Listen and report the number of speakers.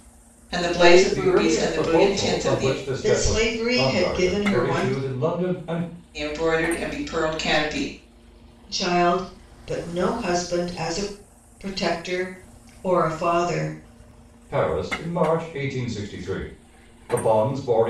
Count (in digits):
3